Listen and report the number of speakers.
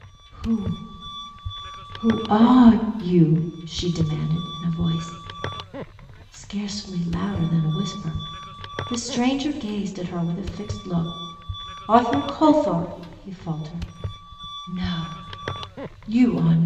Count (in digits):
1